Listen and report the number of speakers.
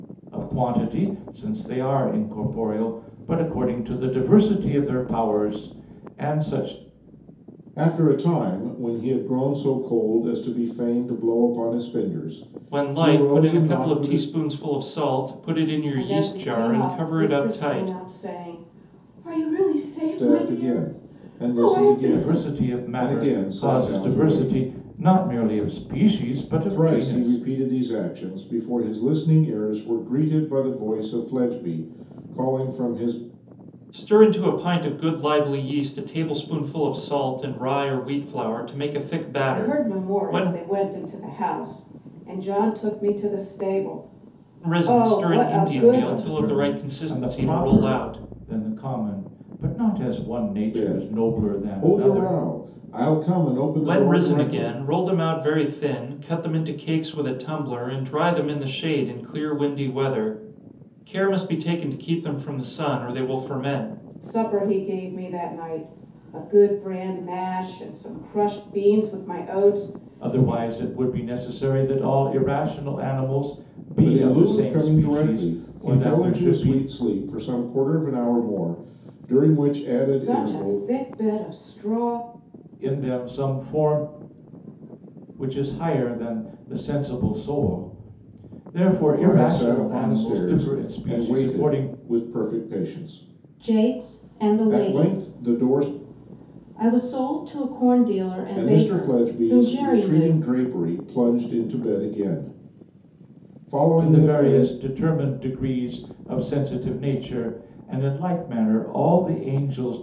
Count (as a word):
four